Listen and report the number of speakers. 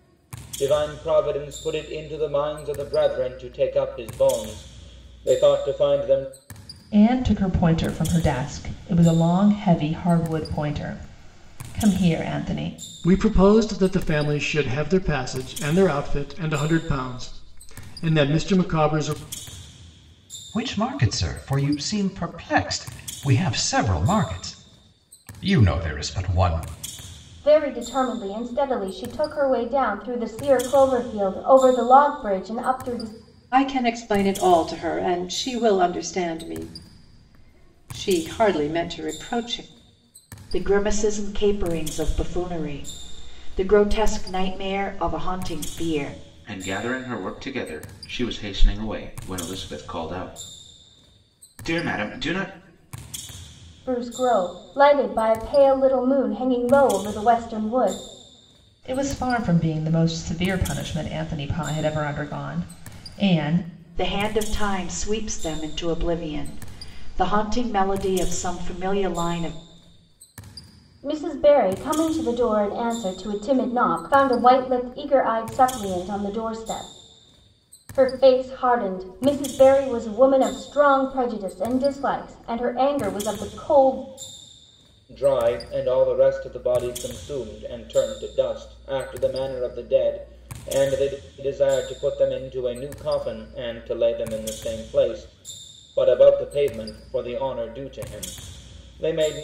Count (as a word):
eight